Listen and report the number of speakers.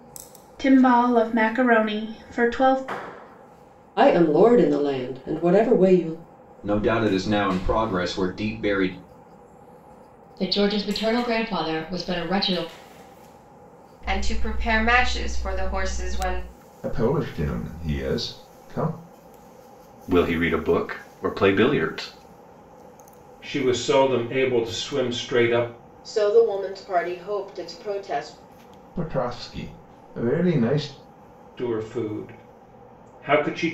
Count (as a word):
nine